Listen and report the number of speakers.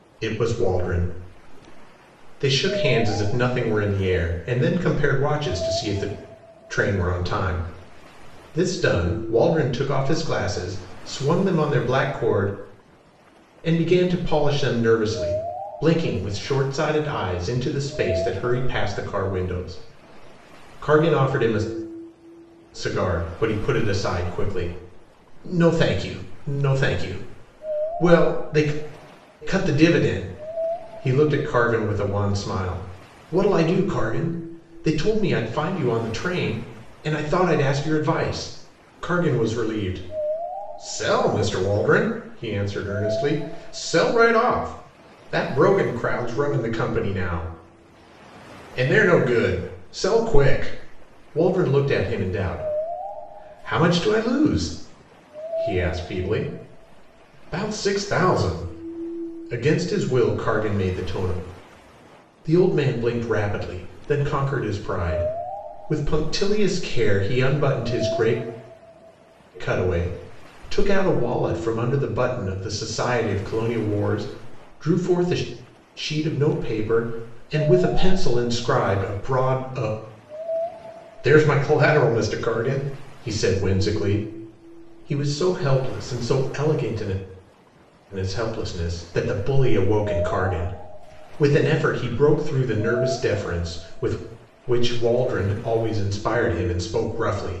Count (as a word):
one